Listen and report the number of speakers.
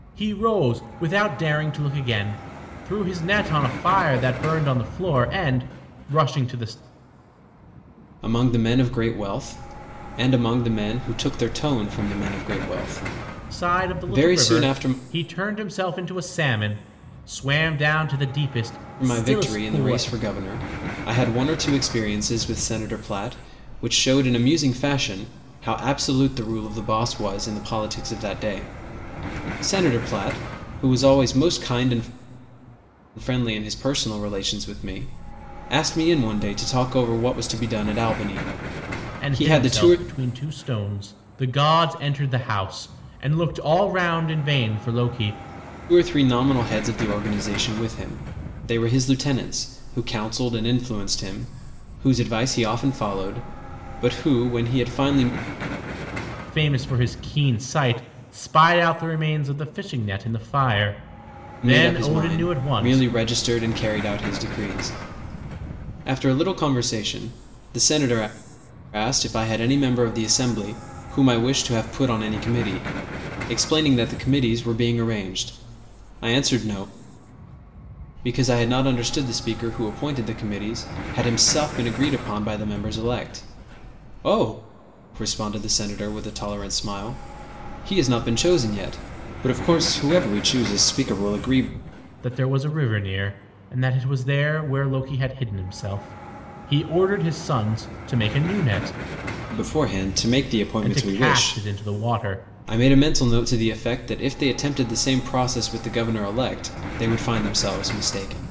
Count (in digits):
2